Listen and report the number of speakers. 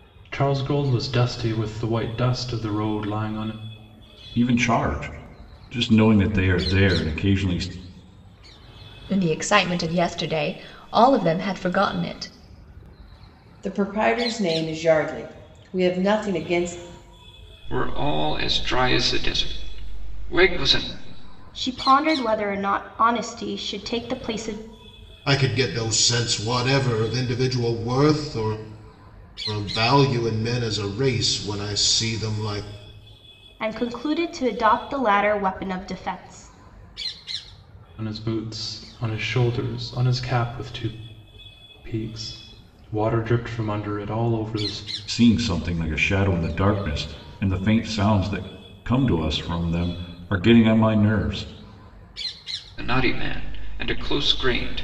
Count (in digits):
7